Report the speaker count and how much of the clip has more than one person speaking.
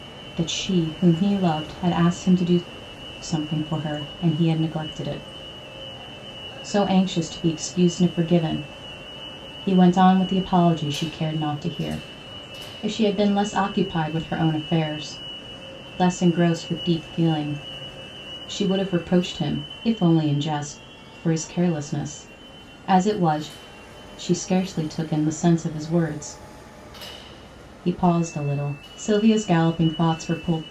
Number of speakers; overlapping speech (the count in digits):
1, no overlap